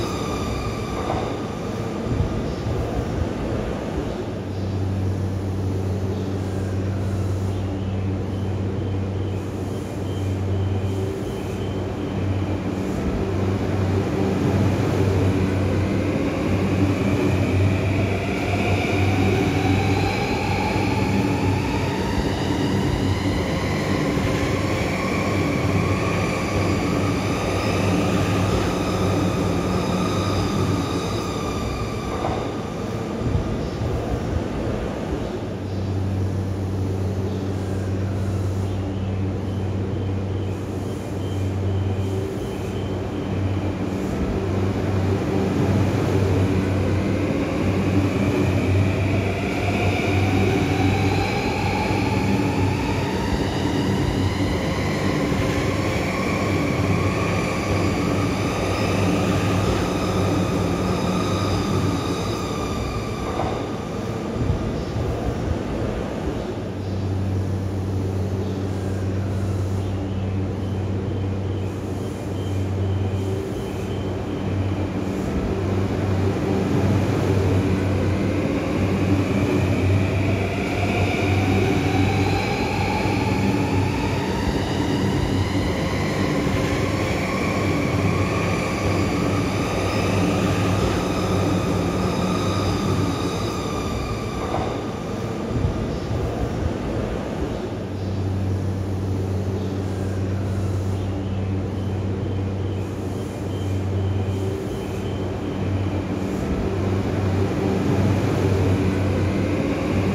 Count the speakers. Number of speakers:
0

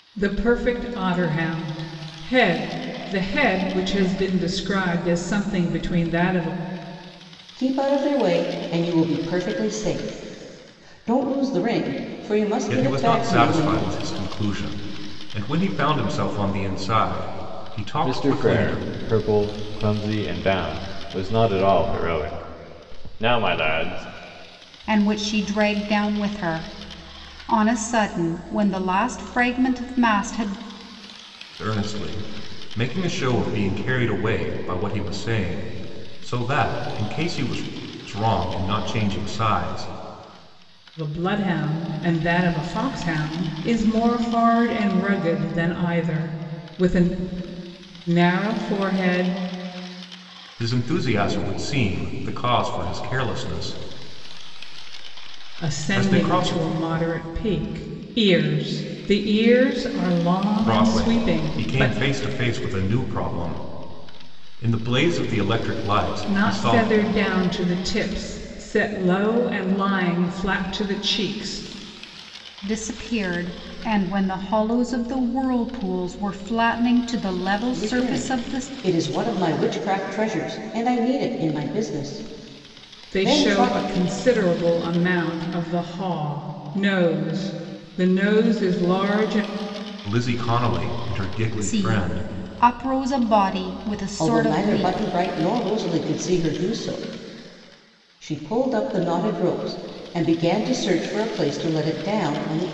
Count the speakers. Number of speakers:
5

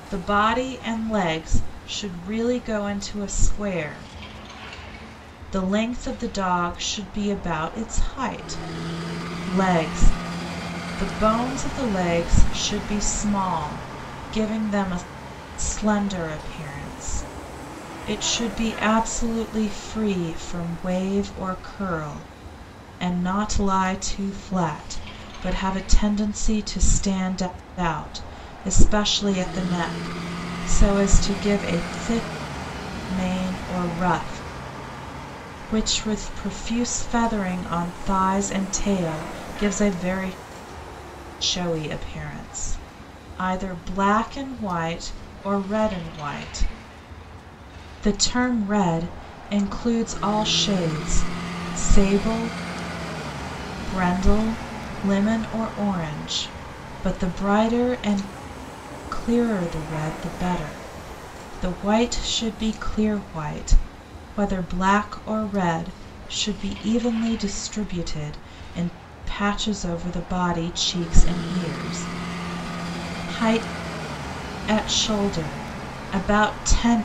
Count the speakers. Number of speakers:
1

